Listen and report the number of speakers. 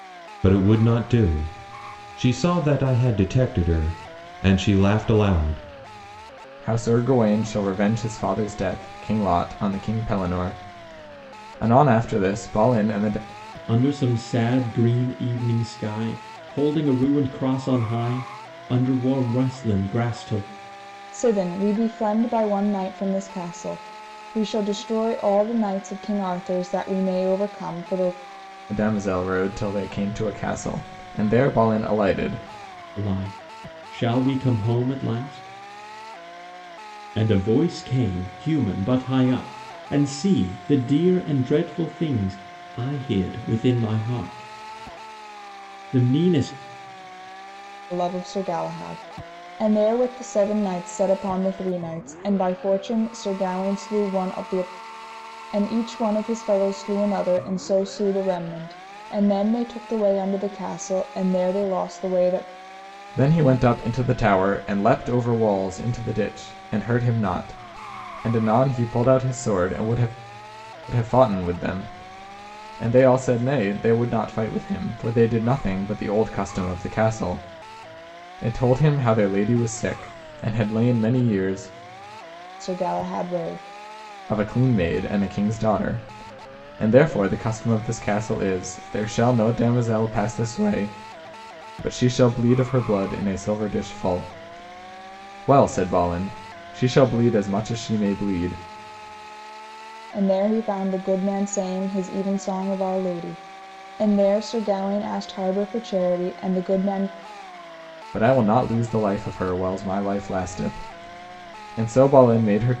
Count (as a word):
four